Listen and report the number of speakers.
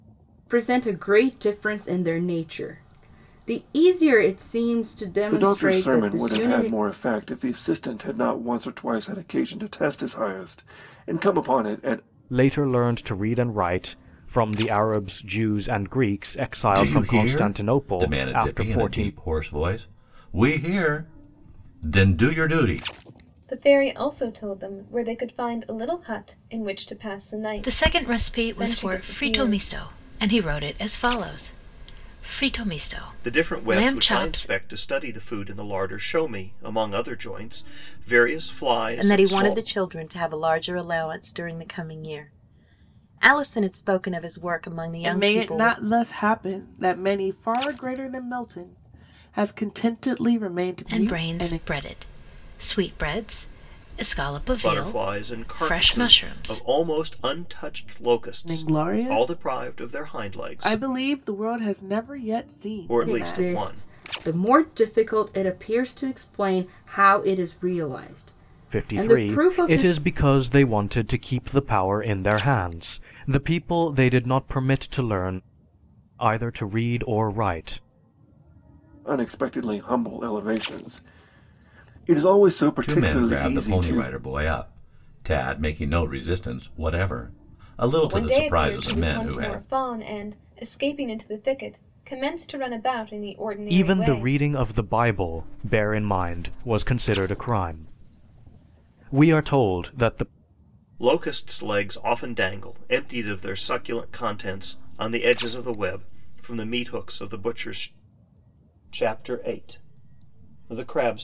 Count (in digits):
9